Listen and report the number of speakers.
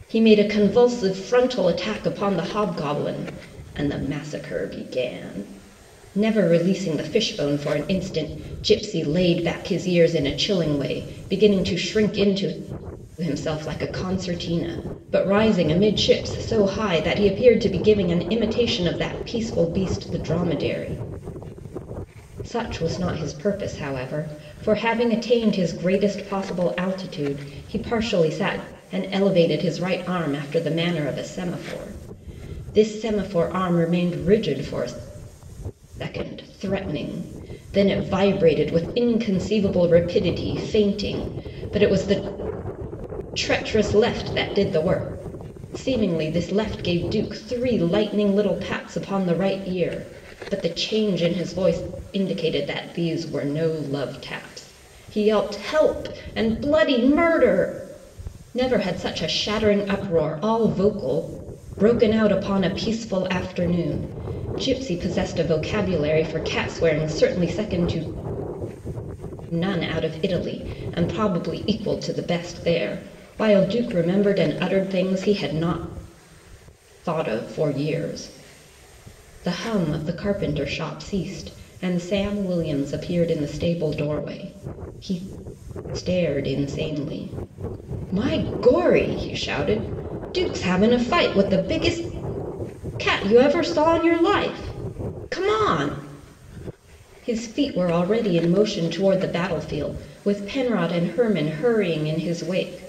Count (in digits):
1